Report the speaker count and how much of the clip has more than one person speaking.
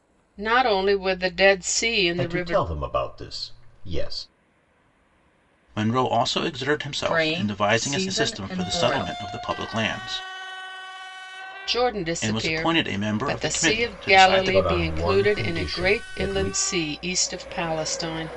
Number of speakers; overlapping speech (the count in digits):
4, about 39%